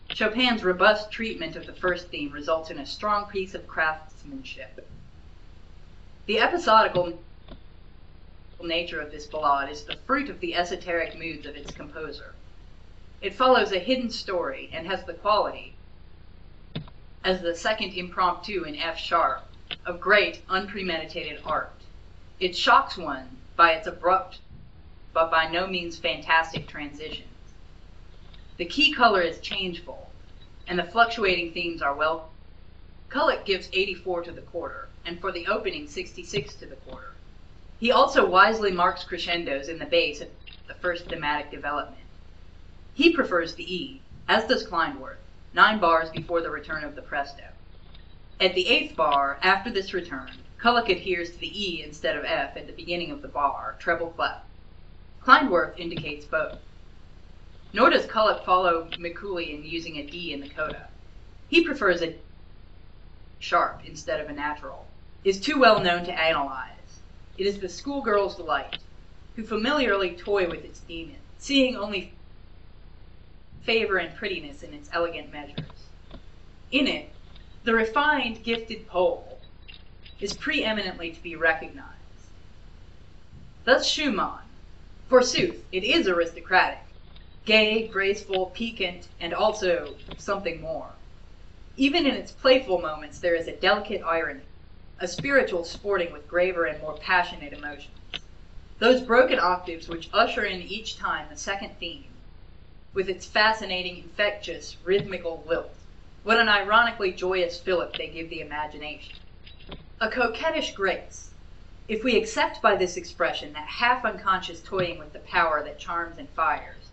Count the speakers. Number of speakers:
one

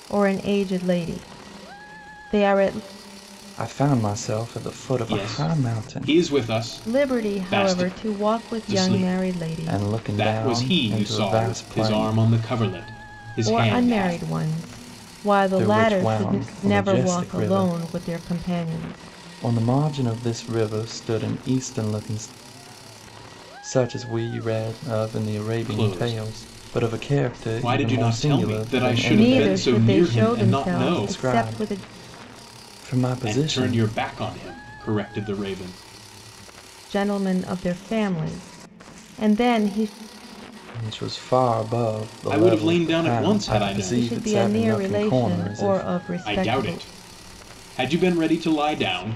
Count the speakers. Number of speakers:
three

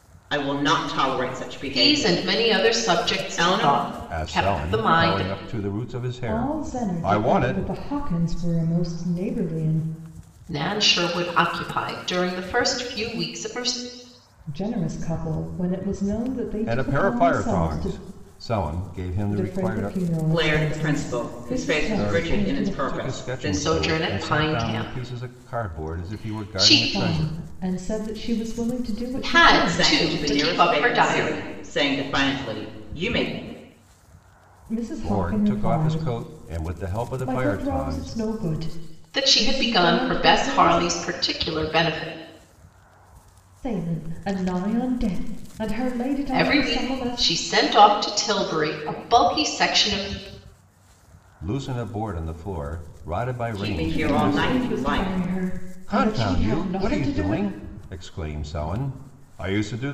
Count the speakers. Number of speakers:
four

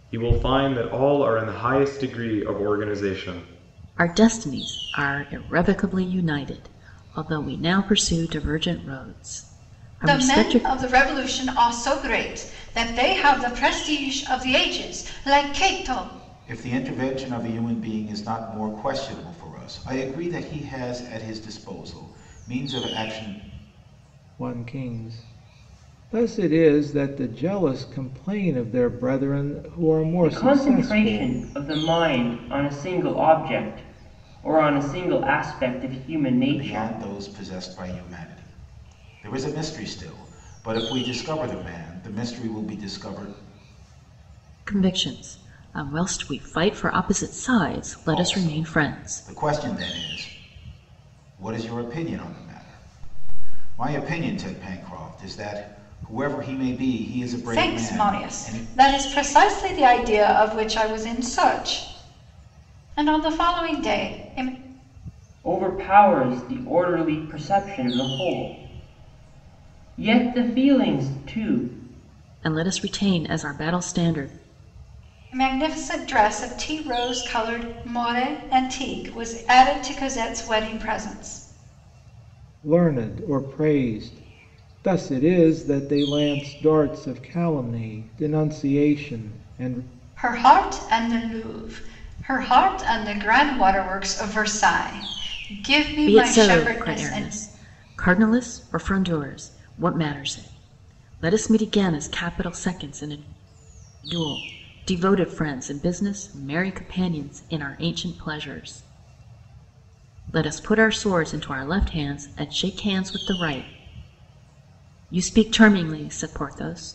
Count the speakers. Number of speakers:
six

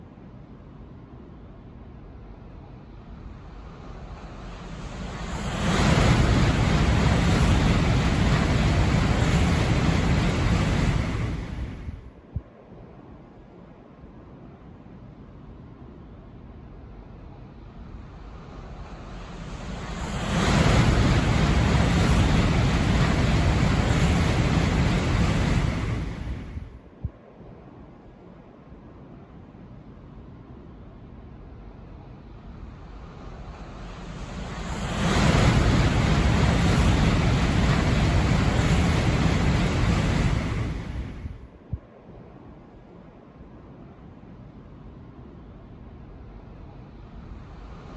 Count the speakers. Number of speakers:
zero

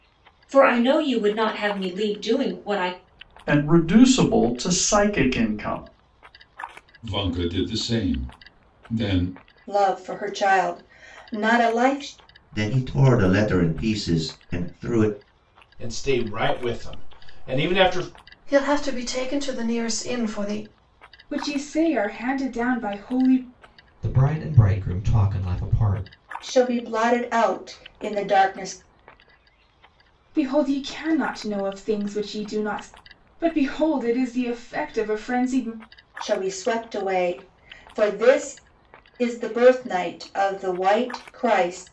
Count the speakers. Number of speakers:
nine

